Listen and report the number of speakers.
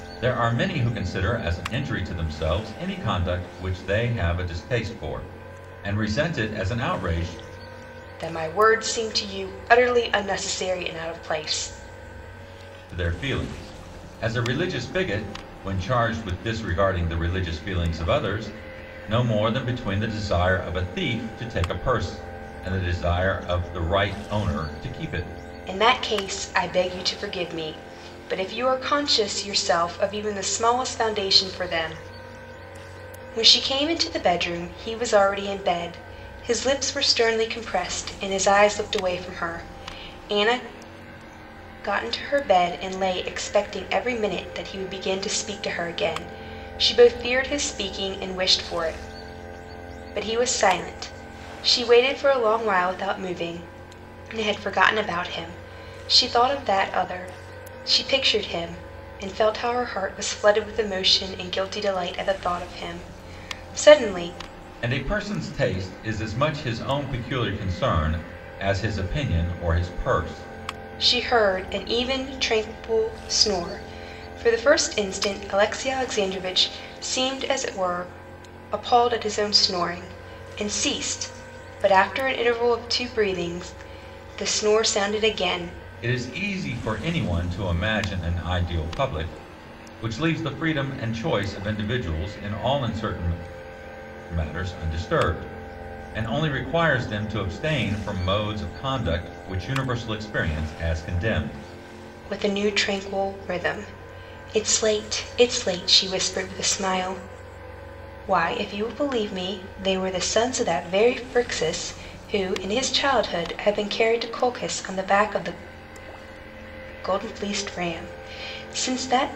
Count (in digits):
2